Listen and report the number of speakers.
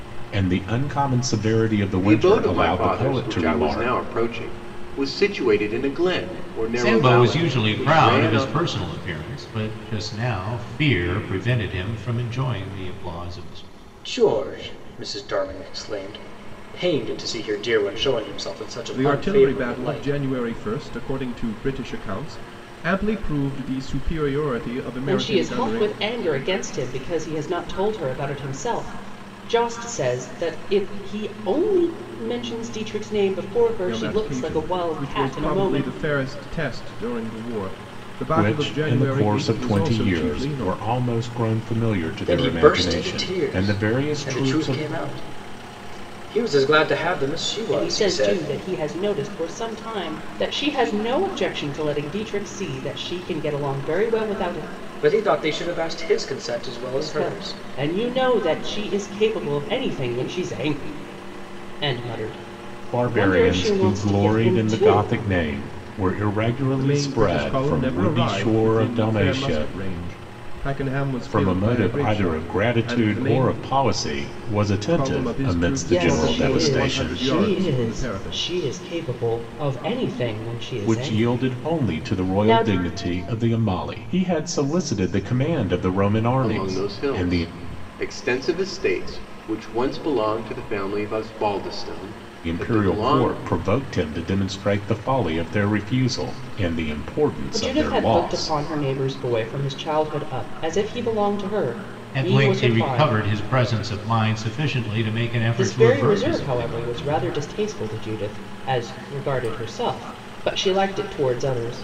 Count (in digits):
6